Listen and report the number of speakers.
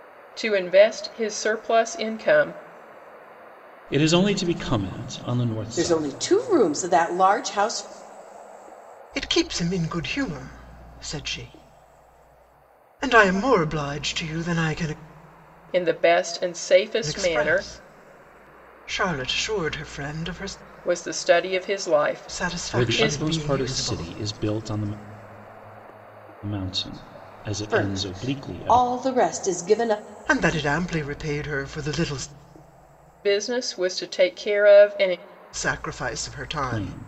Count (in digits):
4